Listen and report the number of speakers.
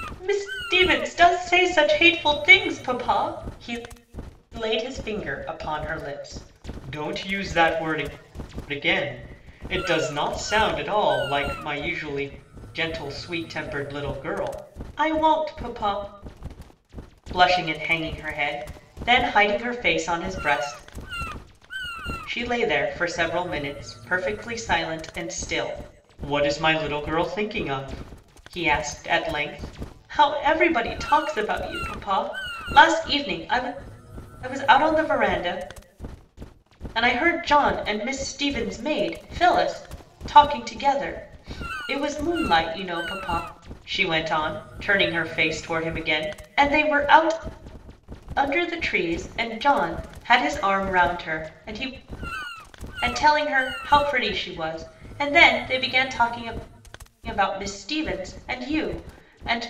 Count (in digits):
1